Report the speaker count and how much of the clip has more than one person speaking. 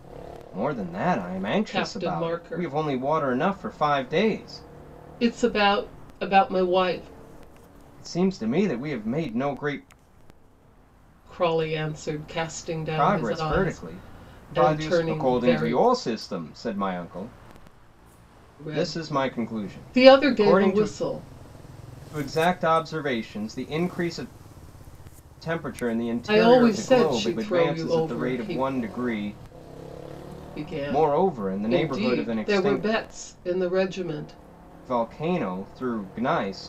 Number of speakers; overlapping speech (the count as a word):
two, about 27%